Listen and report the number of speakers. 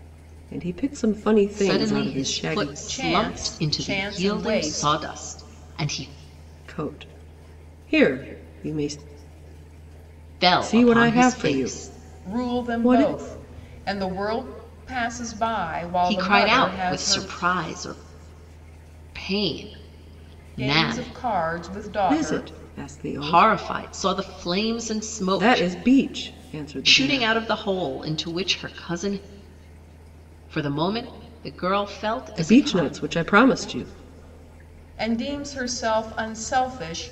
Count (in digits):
3